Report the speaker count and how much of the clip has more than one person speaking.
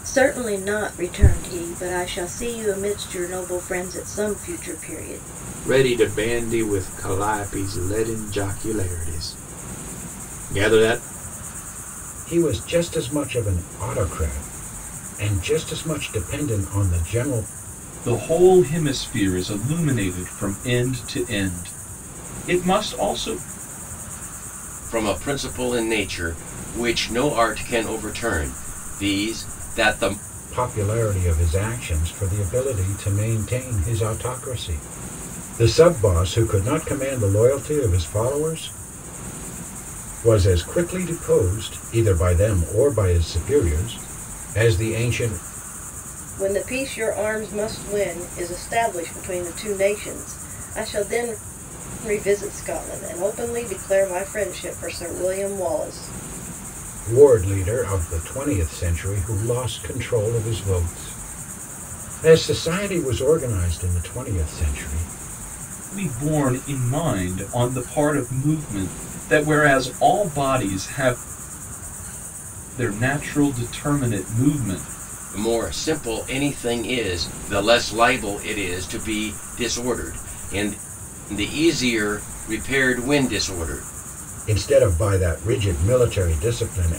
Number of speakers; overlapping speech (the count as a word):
five, no overlap